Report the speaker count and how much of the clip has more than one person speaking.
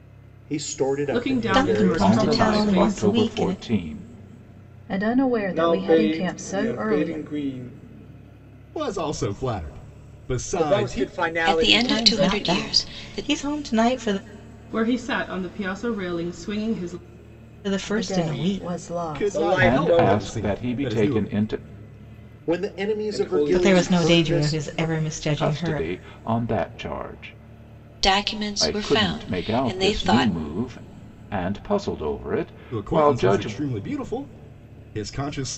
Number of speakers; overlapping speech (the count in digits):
9, about 43%